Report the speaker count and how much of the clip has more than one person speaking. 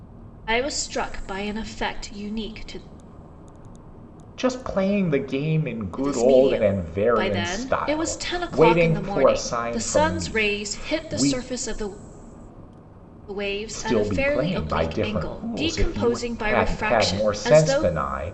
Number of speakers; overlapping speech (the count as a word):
two, about 50%